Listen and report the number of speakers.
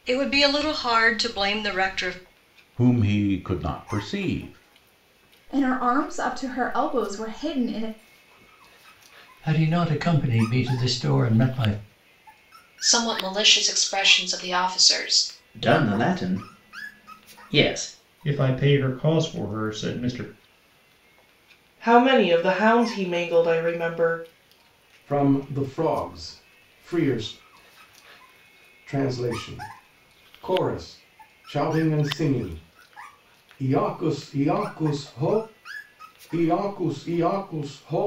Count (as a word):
nine